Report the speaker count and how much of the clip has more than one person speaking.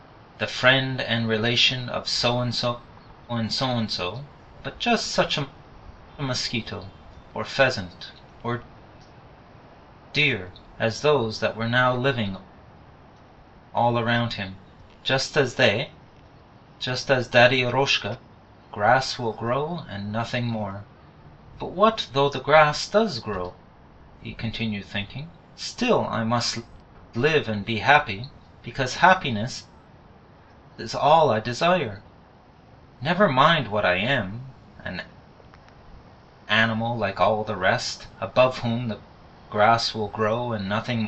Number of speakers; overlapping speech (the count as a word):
one, no overlap